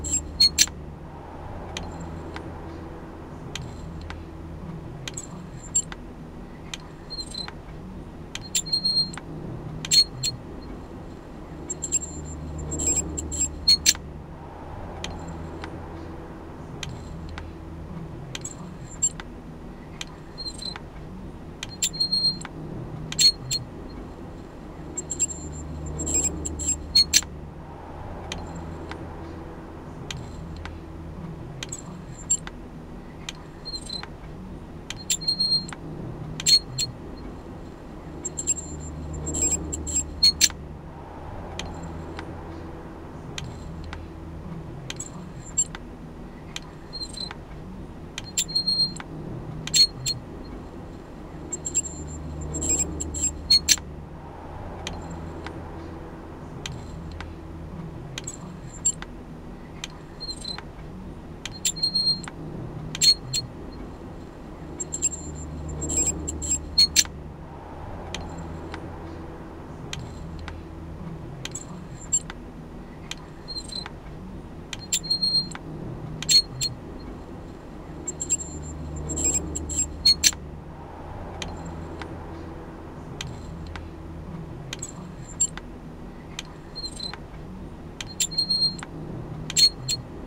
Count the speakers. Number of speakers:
zero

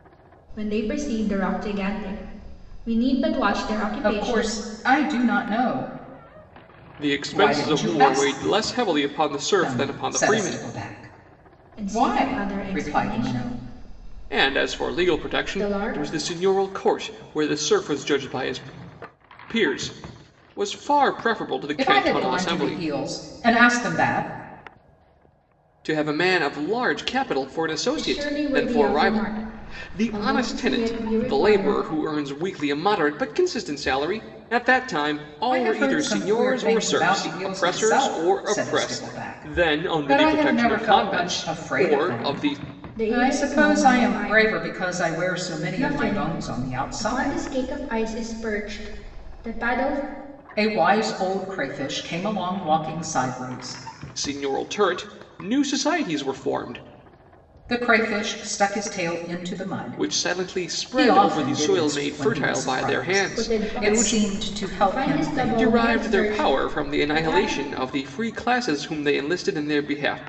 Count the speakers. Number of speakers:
three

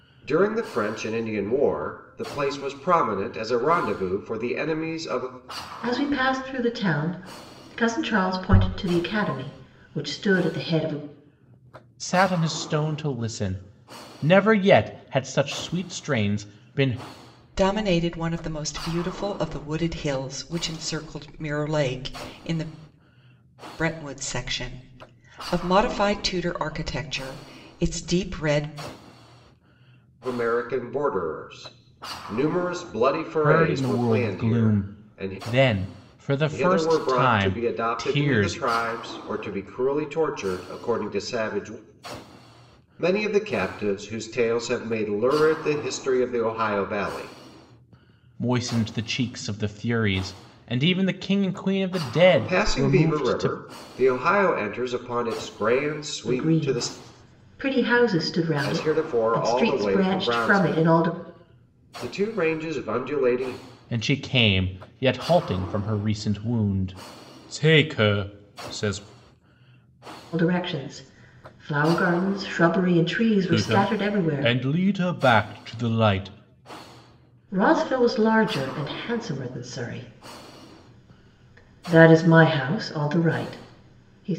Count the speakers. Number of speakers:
four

